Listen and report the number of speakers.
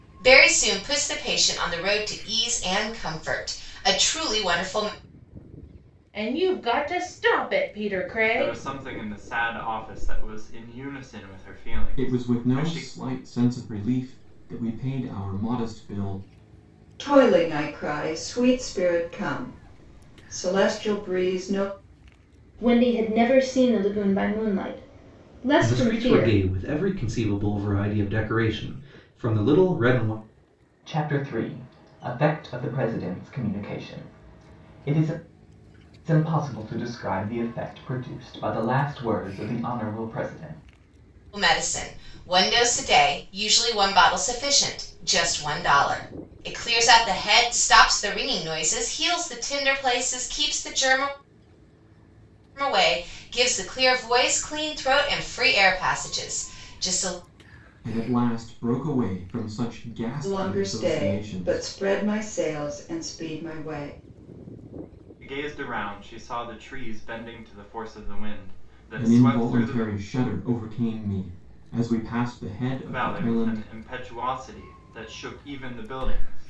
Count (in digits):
8